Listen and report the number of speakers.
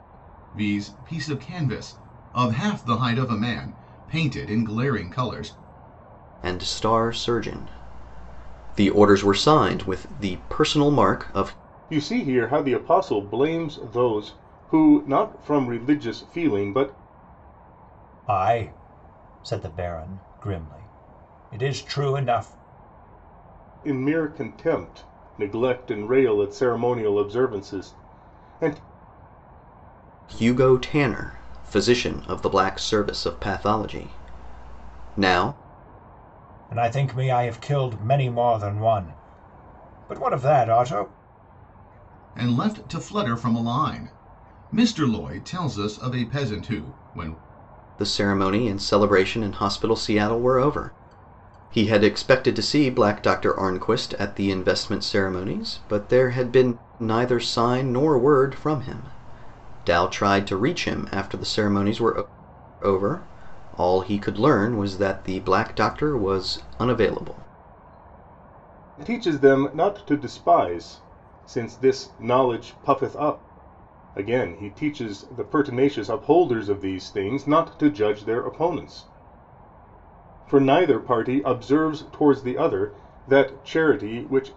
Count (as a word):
four